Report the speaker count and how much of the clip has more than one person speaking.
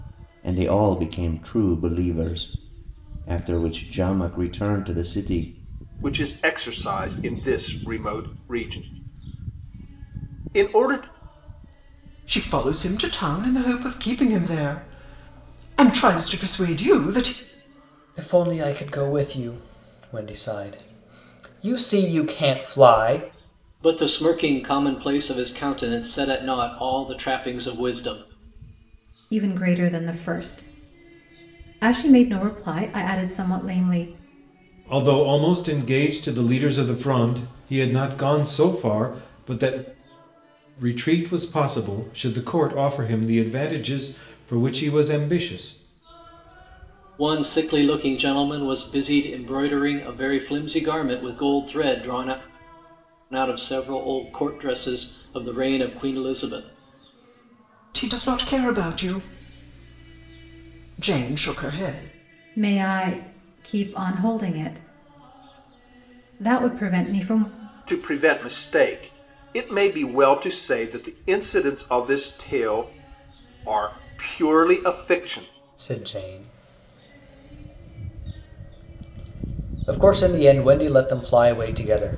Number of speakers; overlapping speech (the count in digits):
7, no overlap